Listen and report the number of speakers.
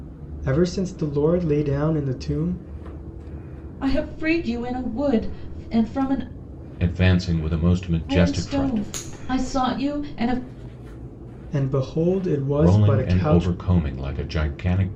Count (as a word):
three